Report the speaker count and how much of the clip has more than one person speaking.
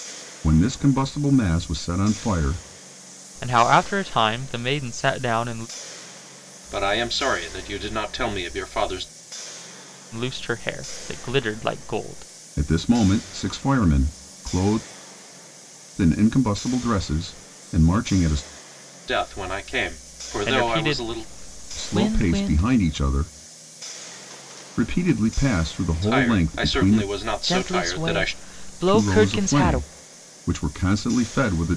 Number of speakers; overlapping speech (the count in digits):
3, about 16%